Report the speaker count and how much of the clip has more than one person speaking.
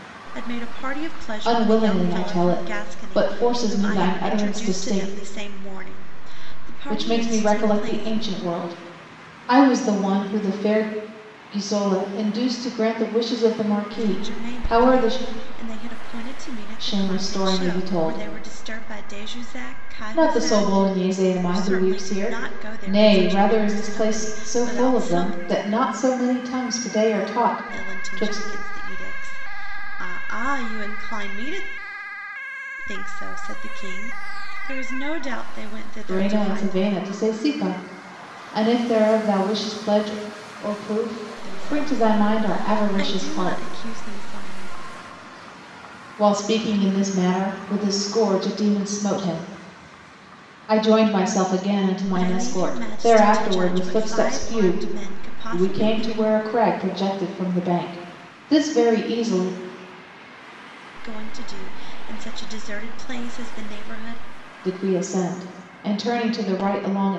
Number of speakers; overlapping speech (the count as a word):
two, about 29%